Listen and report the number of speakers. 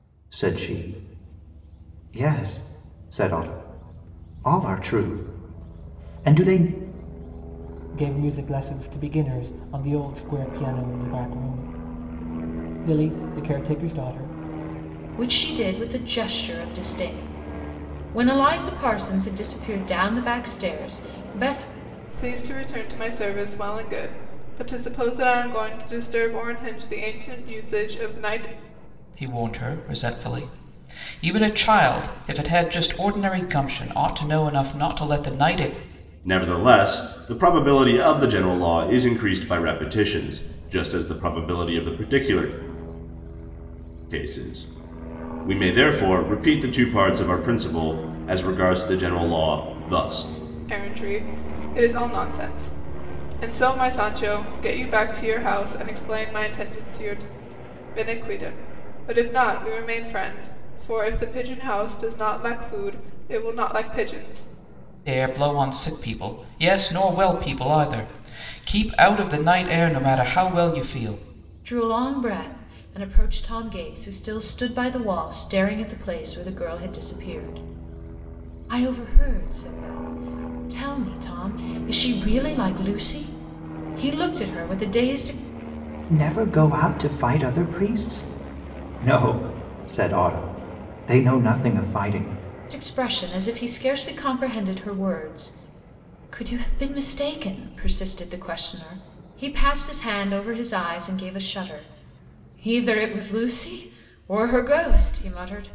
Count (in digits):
6